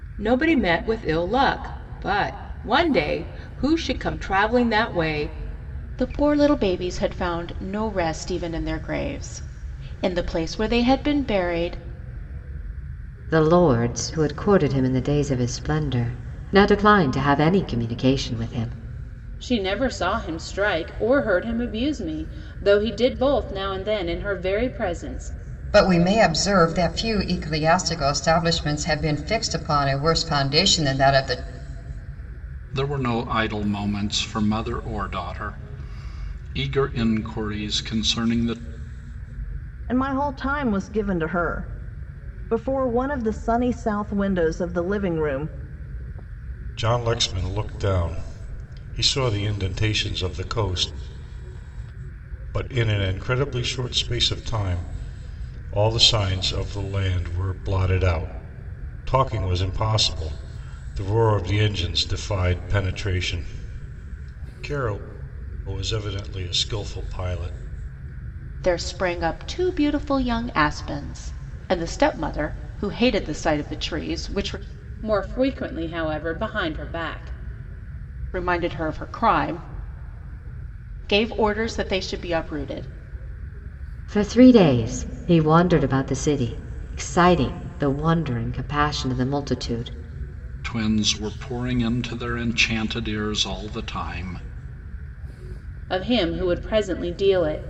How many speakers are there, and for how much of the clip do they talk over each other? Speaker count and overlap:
eight, no overlap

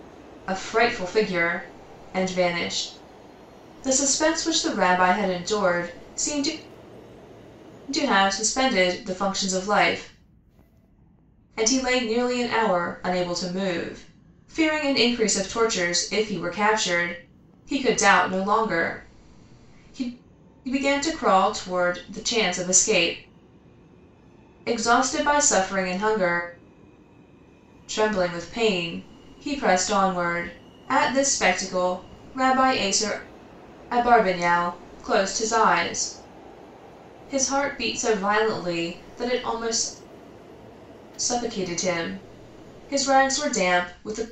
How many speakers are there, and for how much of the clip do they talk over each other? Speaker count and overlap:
one, no overlap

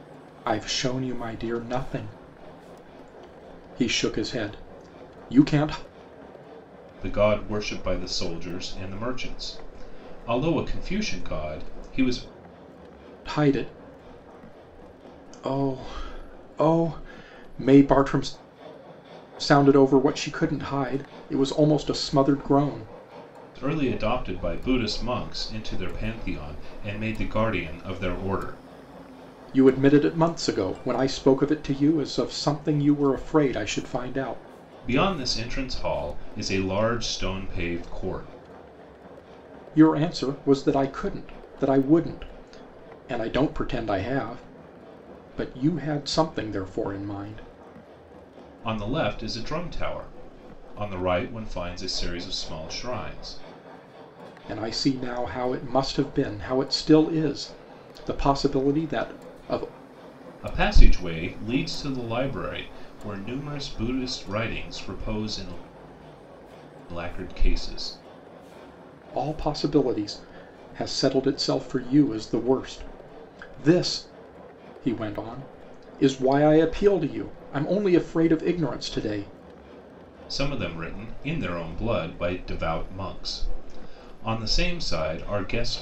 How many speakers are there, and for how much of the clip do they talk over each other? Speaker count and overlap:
two, no overlap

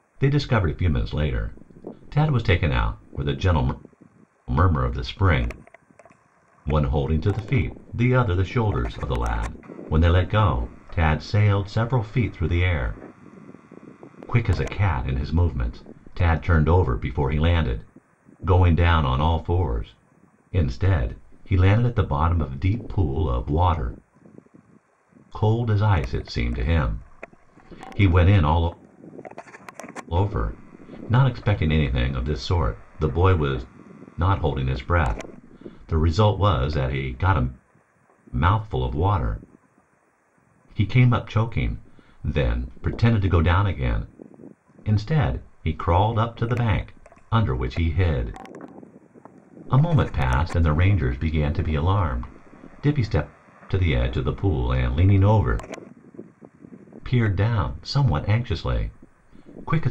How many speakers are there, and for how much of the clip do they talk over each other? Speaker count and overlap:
one, no overlap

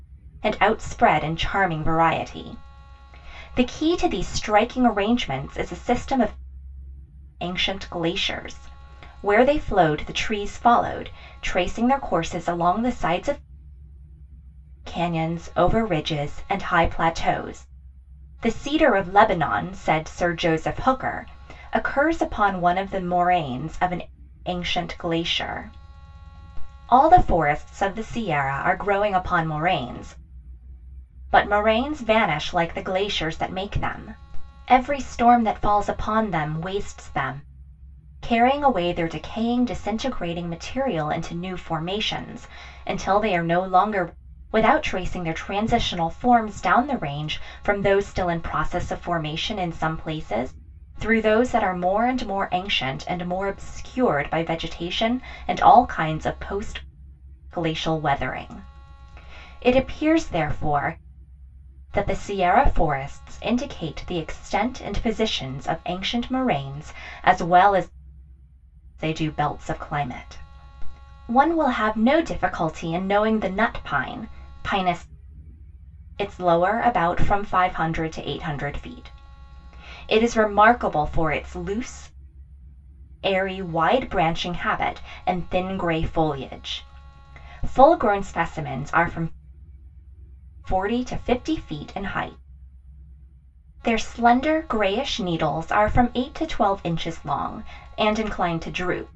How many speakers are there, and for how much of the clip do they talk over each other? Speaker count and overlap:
one, no overlap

